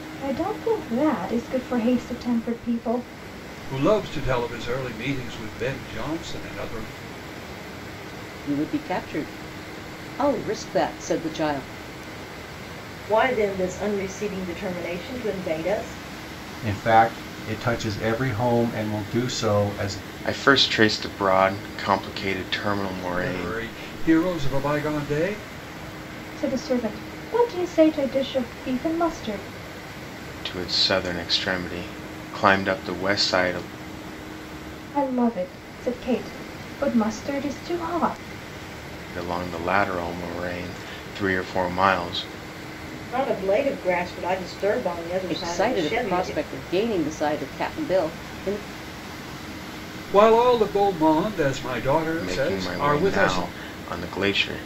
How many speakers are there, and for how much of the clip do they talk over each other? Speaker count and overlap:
six, about 5%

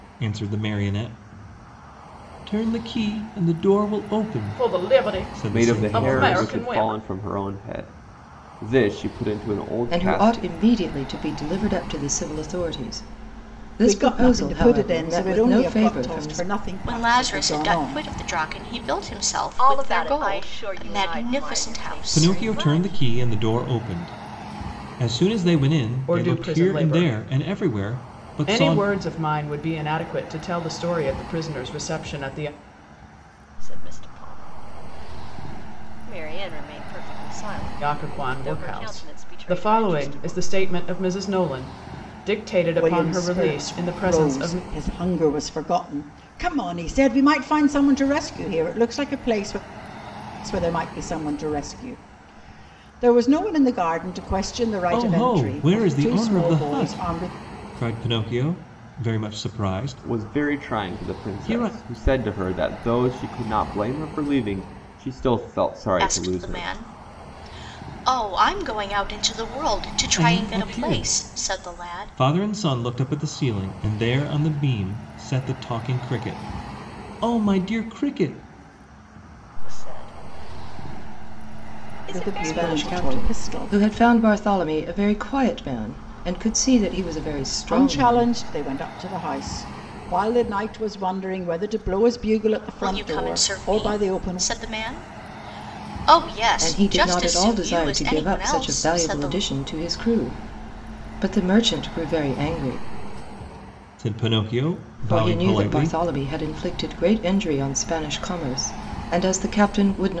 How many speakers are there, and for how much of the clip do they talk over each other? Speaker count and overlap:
seven, about 30%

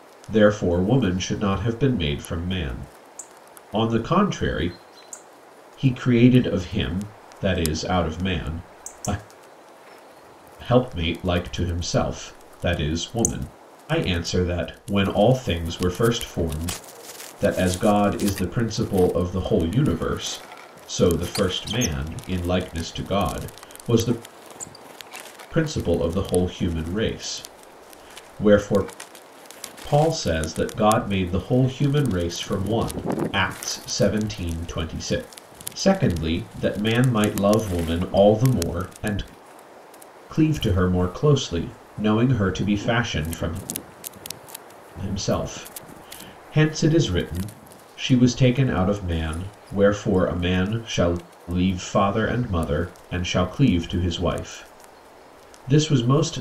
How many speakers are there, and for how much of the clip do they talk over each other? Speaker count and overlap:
one, no overlap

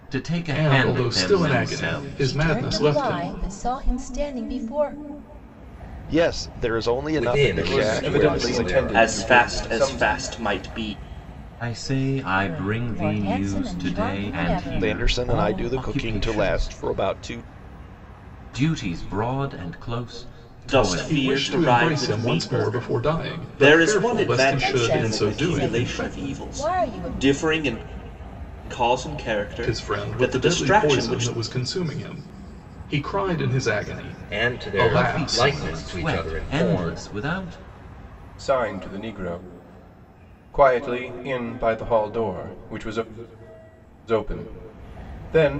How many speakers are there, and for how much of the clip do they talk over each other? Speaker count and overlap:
seven, about 46%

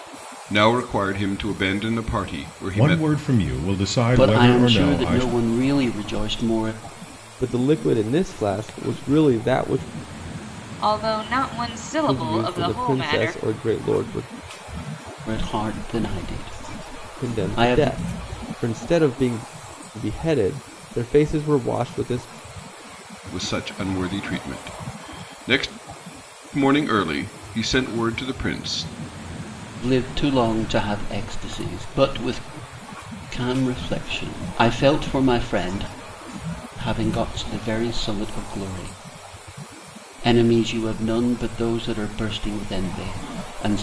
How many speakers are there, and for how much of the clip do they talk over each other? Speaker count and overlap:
five, about 8%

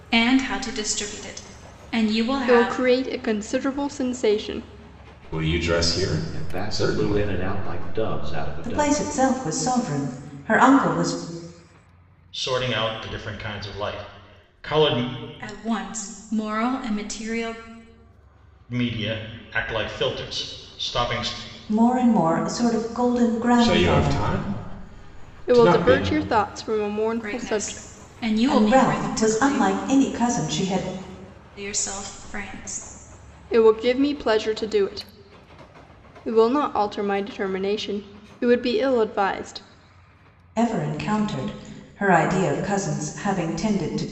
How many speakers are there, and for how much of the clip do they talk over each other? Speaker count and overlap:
six, about 12%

